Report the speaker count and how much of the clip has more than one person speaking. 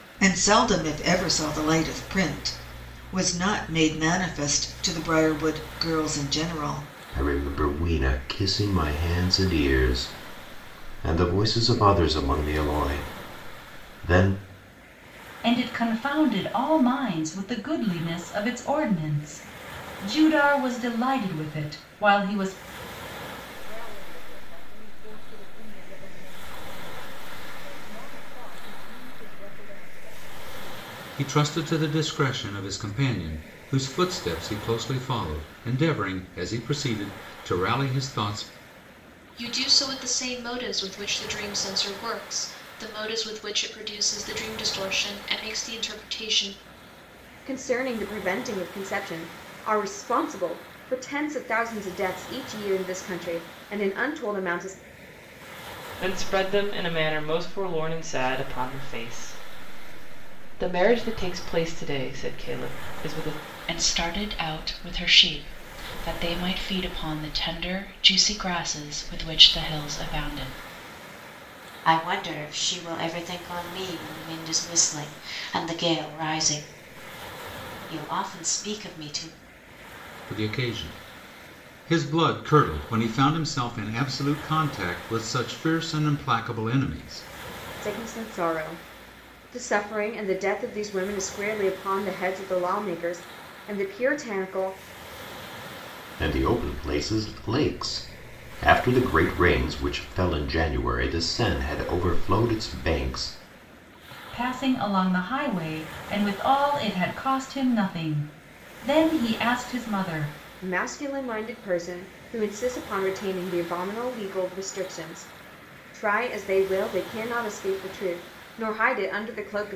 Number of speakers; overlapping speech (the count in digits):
10, no overlap